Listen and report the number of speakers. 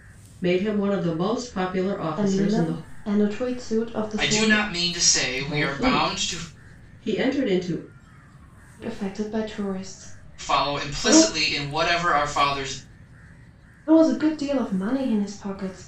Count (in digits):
3